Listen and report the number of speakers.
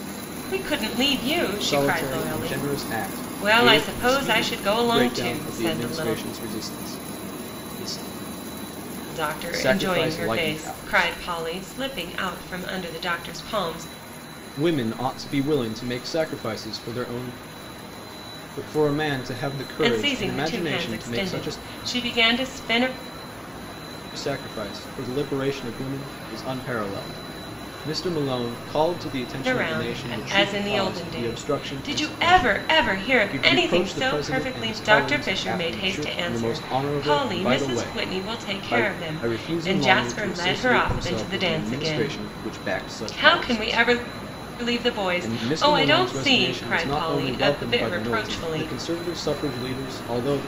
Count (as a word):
two